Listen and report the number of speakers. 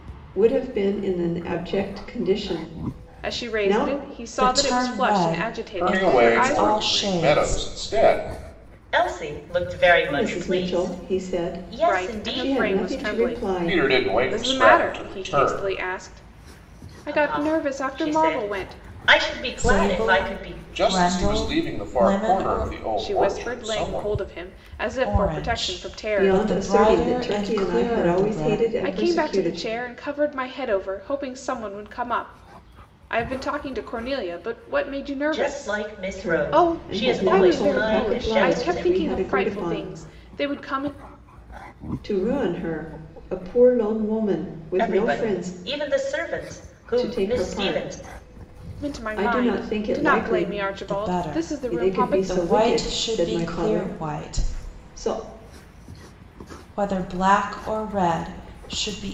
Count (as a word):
five